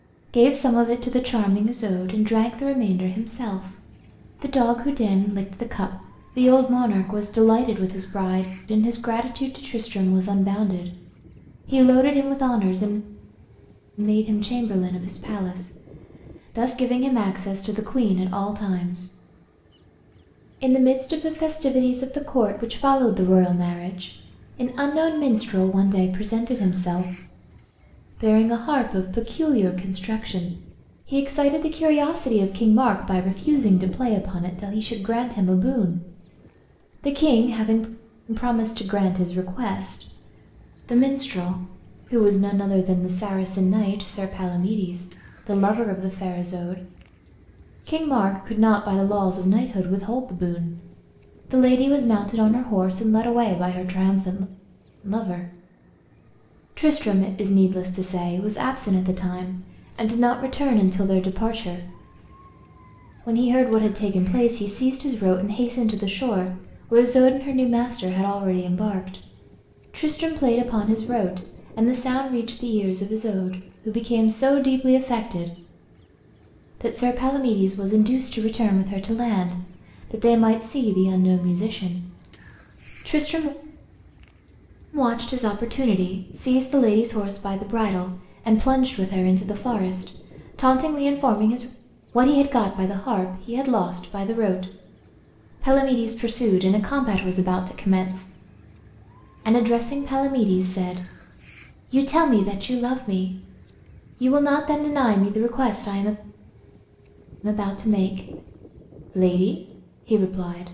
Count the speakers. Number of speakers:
one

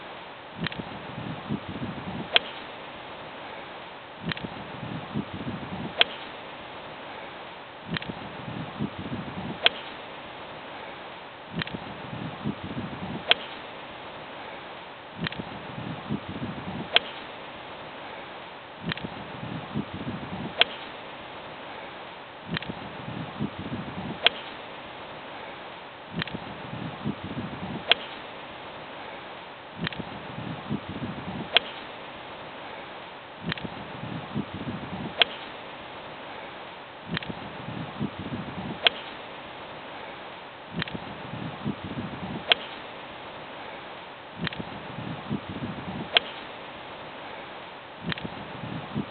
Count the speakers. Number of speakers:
zero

